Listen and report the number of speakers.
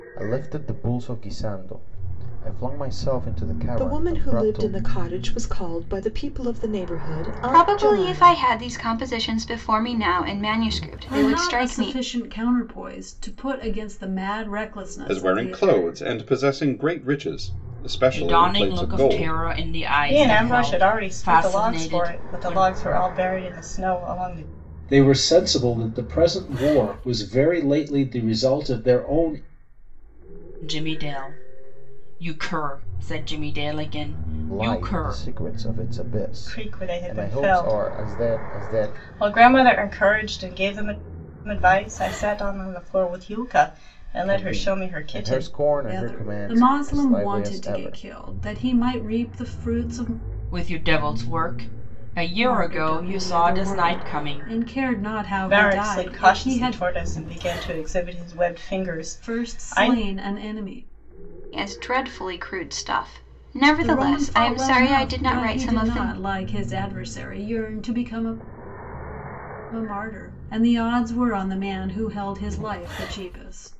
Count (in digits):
8